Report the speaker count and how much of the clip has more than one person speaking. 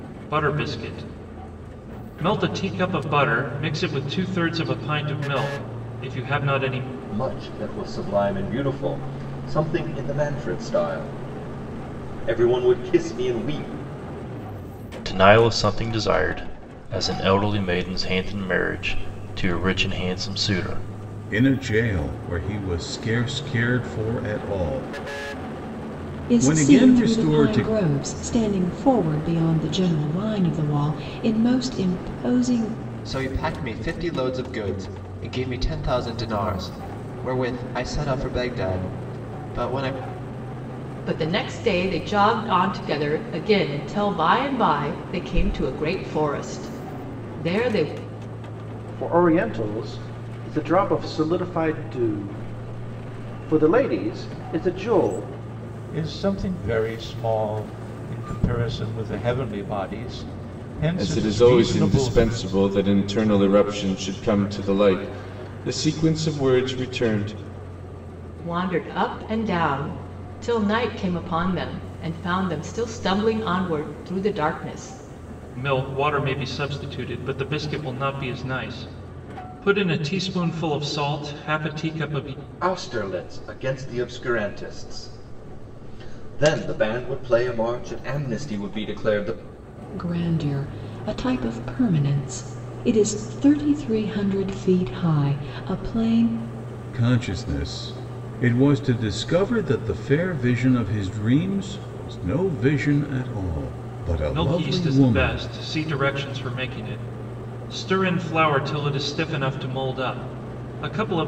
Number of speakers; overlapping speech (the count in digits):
10, about 4%